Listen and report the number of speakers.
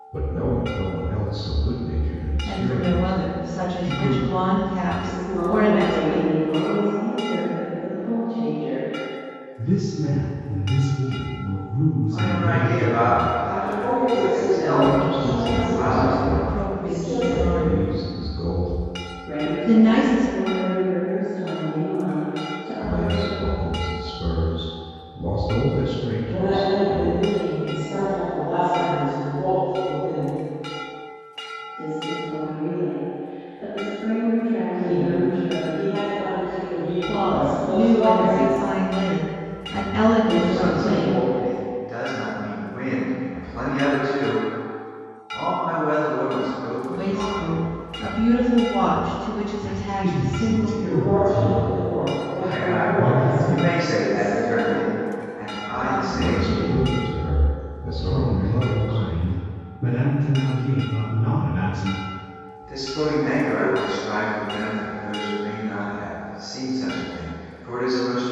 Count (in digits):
6